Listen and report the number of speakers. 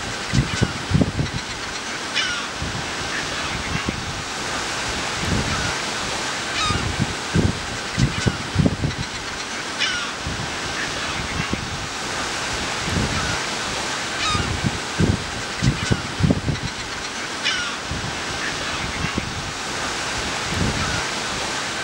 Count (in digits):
0